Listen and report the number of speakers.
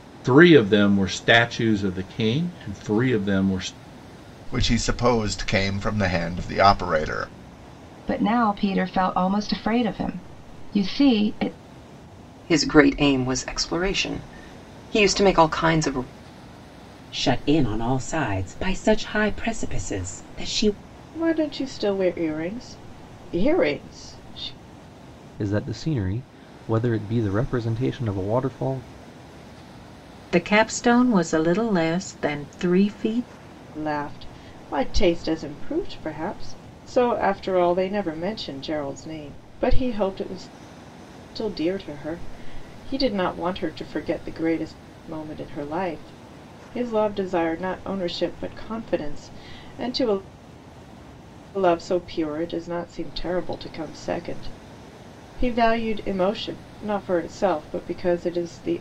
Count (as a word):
eight